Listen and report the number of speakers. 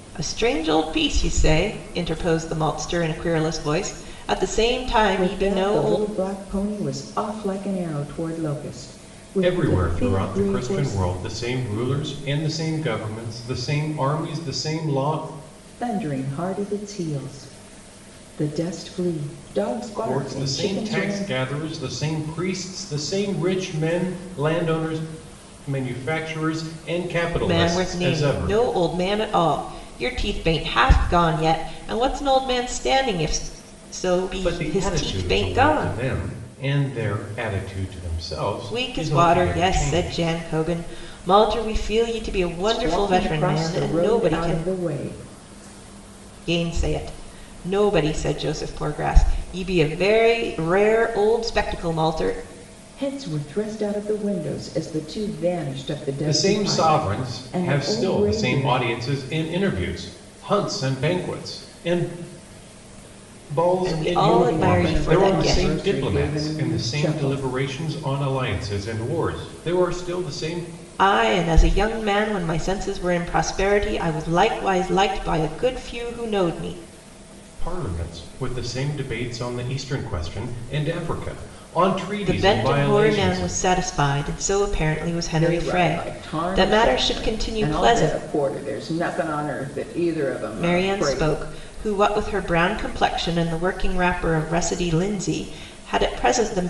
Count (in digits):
3